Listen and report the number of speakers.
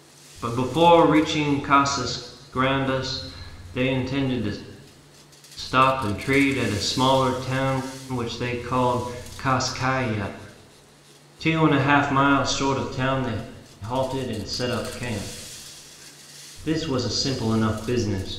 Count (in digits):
1